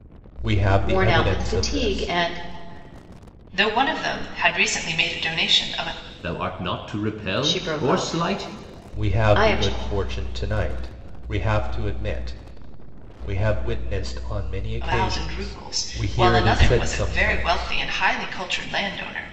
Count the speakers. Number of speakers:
4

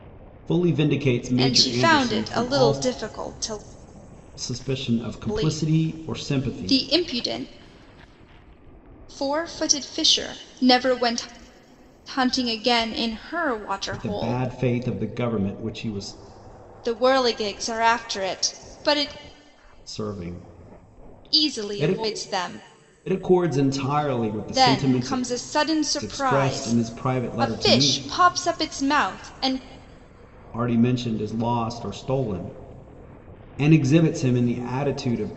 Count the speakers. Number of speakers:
2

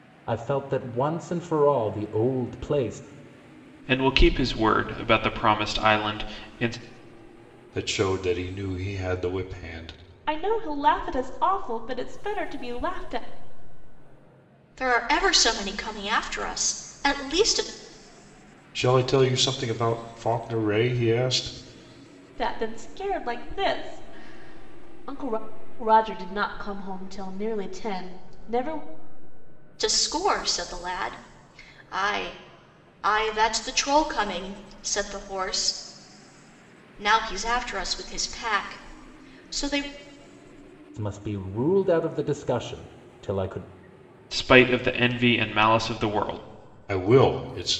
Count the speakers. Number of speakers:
5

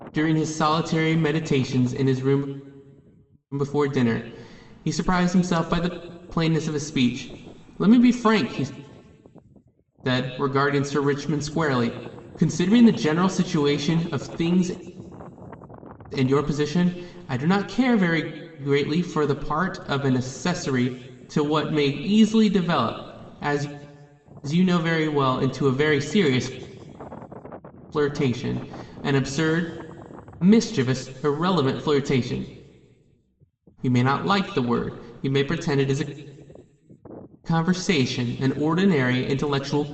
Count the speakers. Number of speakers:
1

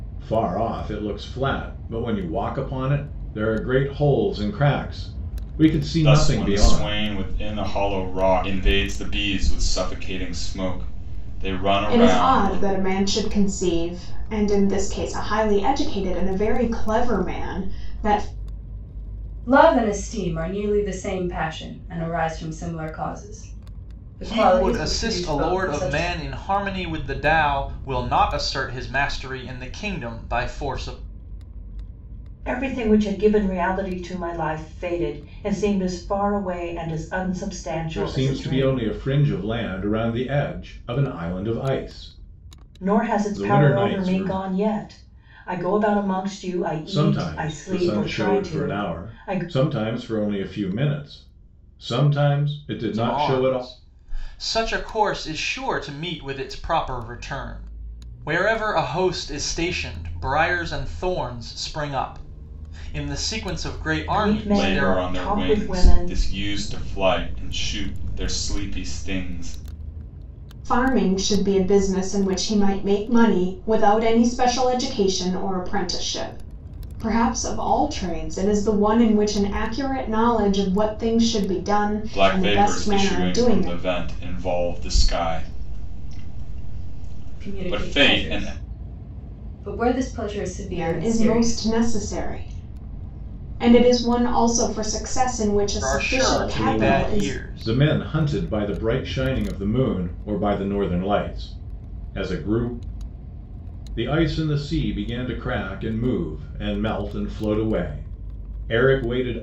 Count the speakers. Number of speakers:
6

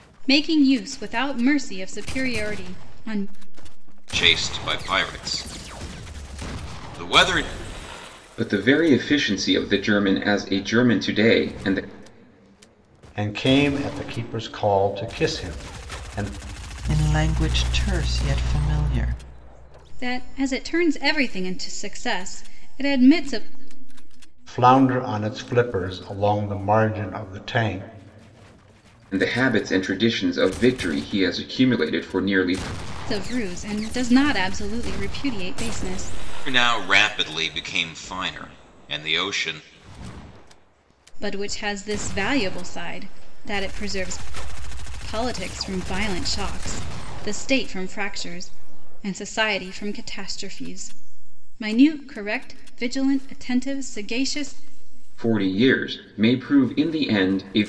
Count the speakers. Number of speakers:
5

